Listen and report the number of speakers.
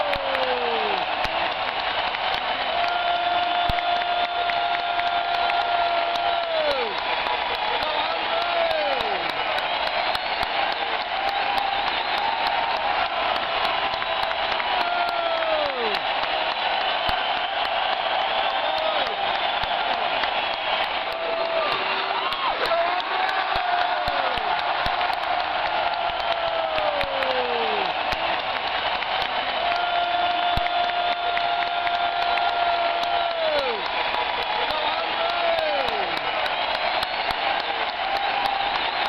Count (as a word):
zero